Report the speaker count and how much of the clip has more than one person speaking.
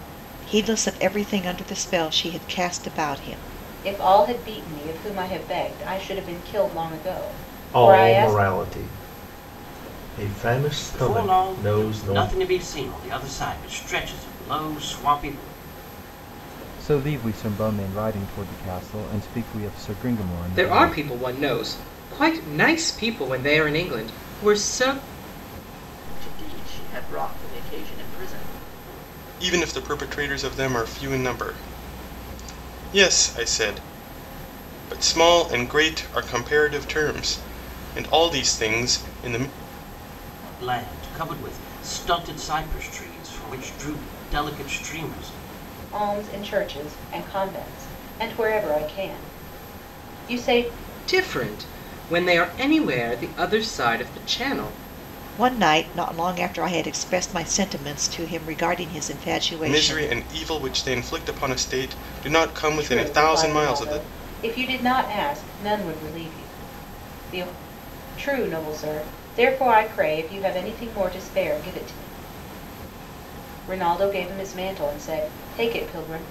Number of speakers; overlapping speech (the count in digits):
8, about 6%